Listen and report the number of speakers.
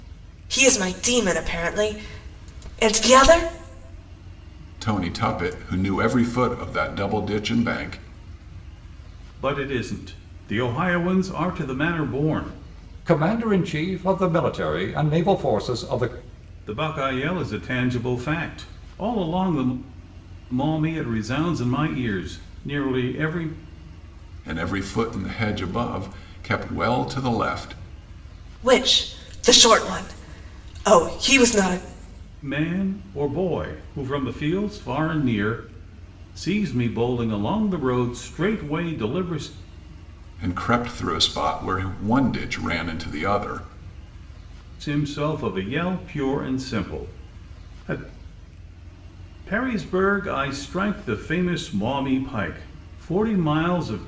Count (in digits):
4